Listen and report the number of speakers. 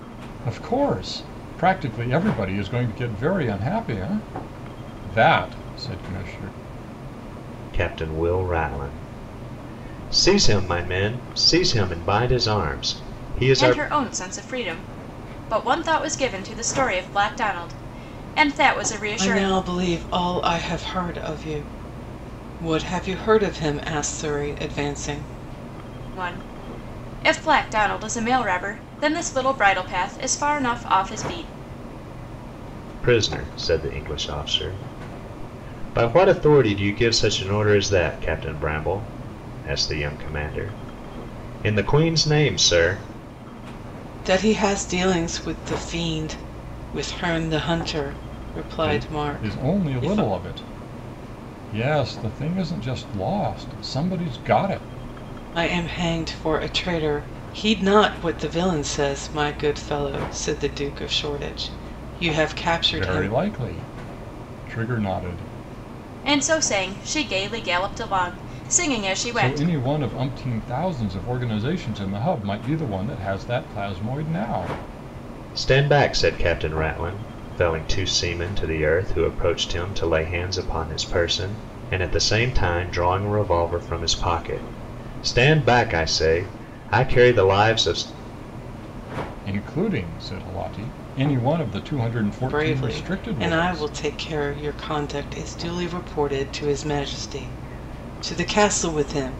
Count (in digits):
4